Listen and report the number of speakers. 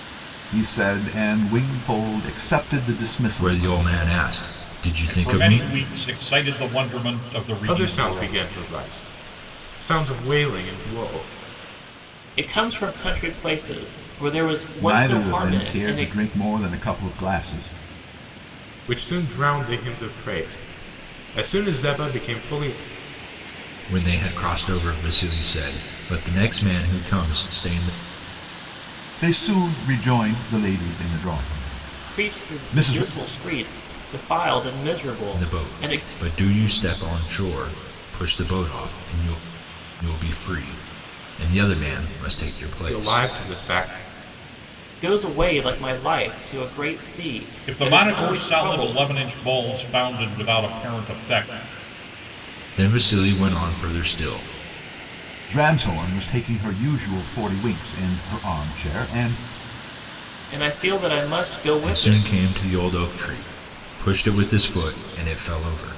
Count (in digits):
5